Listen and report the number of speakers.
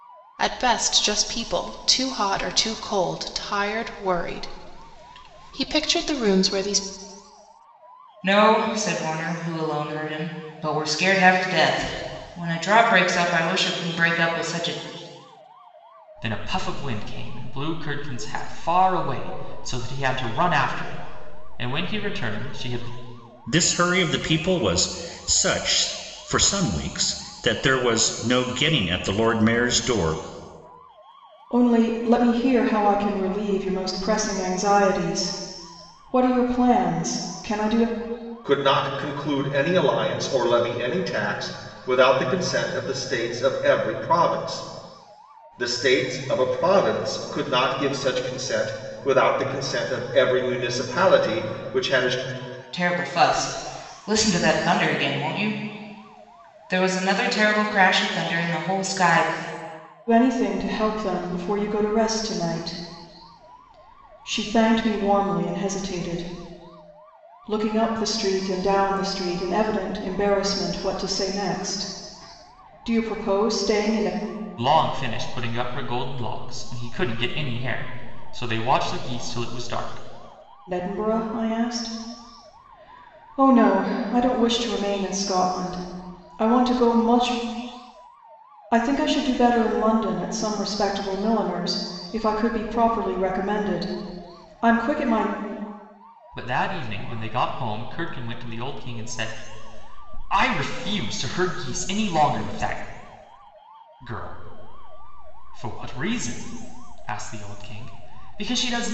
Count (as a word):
six